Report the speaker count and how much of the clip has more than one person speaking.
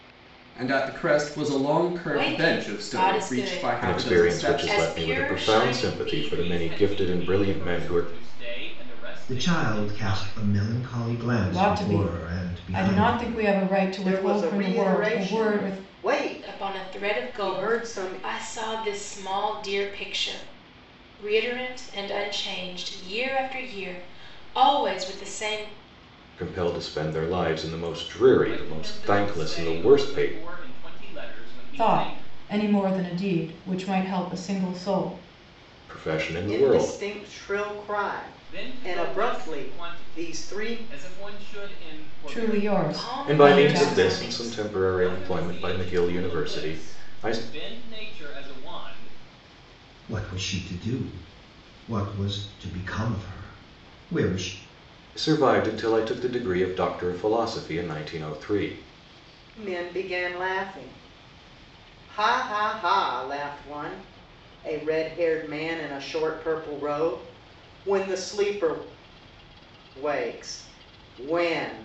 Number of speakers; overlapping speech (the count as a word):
seven, about 33%